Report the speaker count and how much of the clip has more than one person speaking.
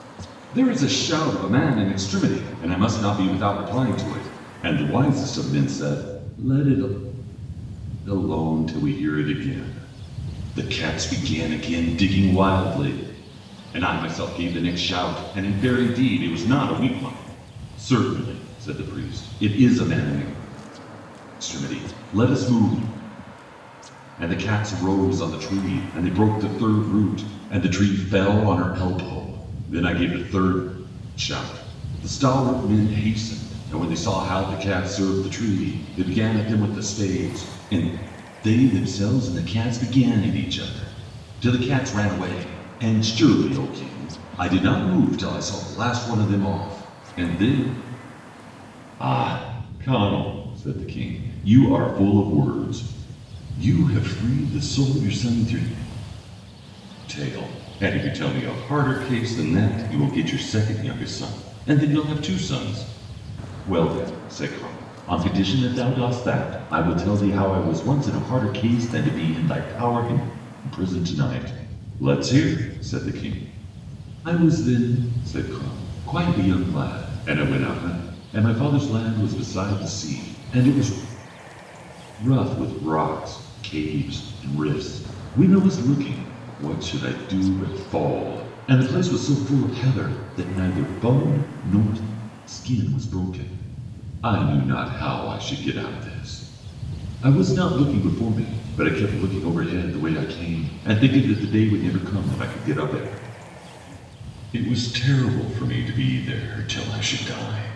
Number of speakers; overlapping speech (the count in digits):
1, no overlap